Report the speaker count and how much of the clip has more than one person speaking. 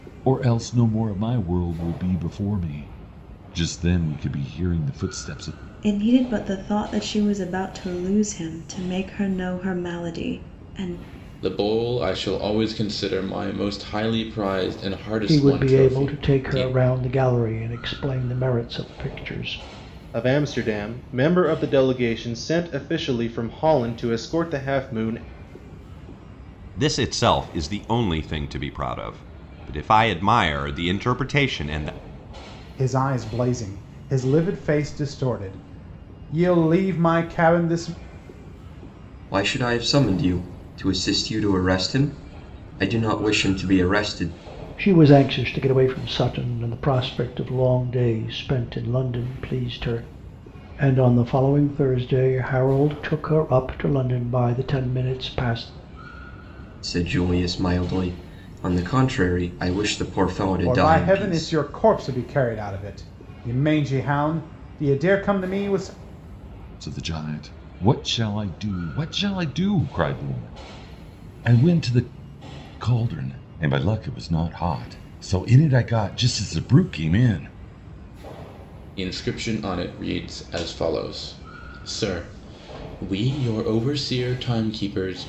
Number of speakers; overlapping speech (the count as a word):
eight, about 3%